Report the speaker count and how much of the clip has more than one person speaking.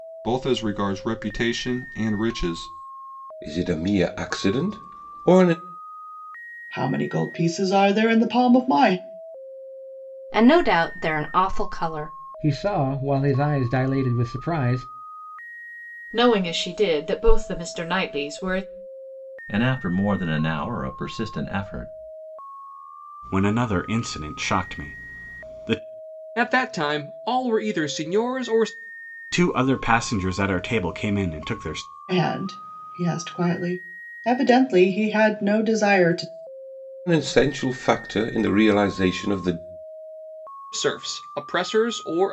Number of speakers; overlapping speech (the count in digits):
9, no overlap